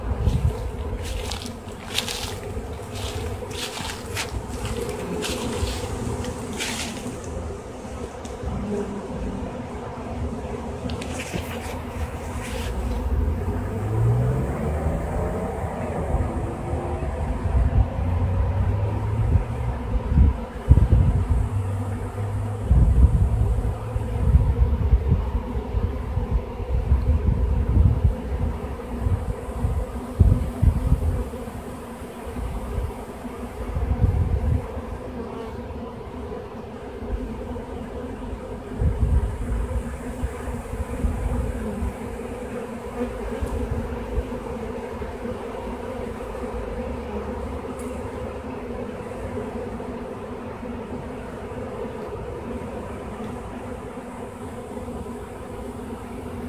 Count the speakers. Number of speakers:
zero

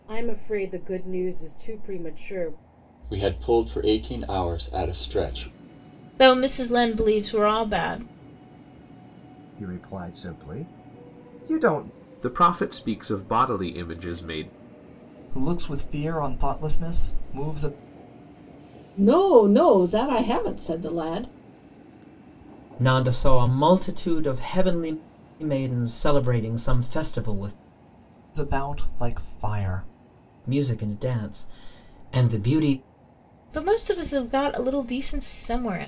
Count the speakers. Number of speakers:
eight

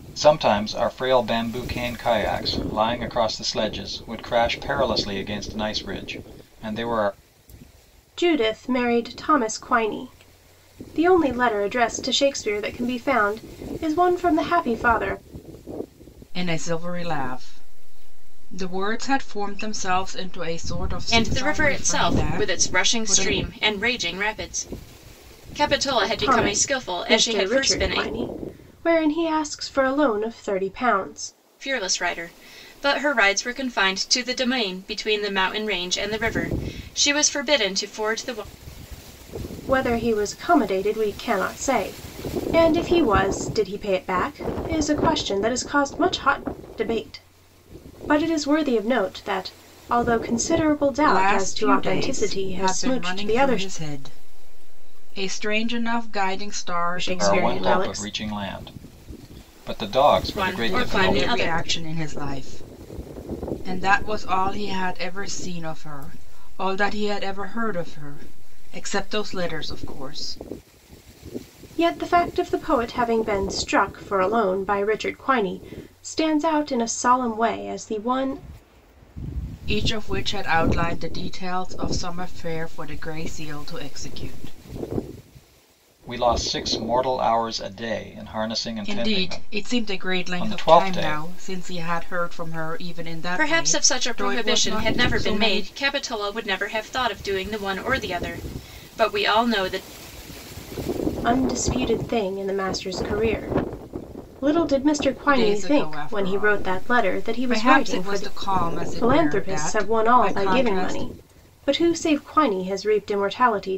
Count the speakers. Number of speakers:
four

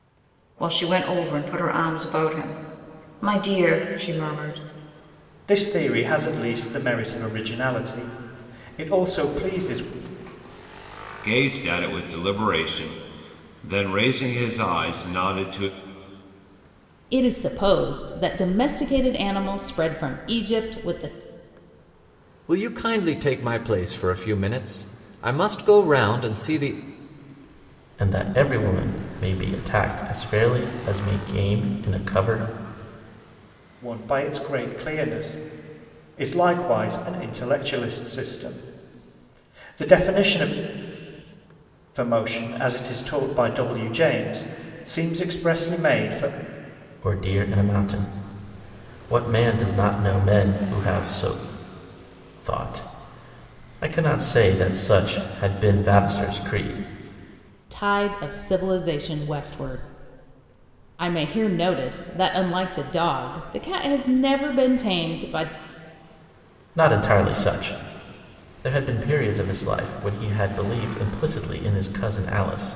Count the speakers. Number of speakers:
six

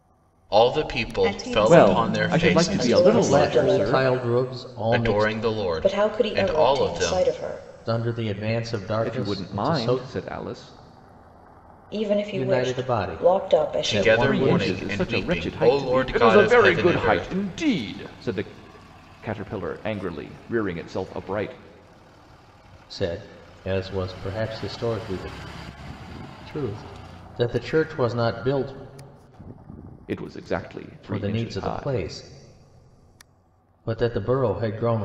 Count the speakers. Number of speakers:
five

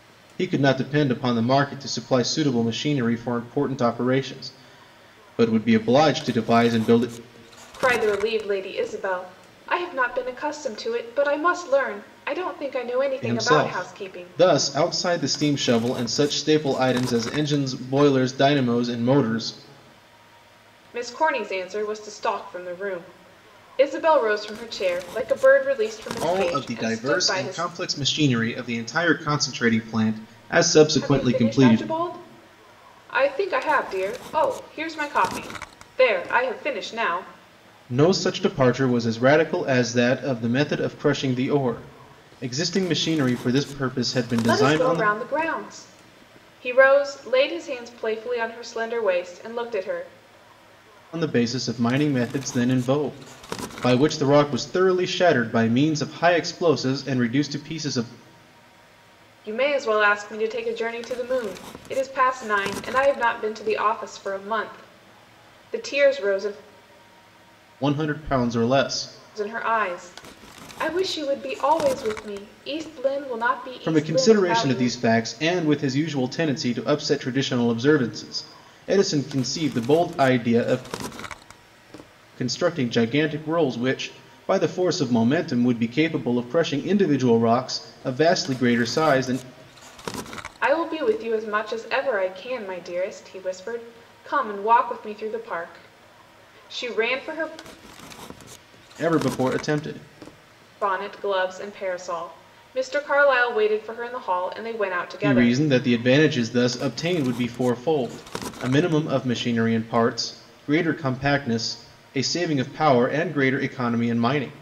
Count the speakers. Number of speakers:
two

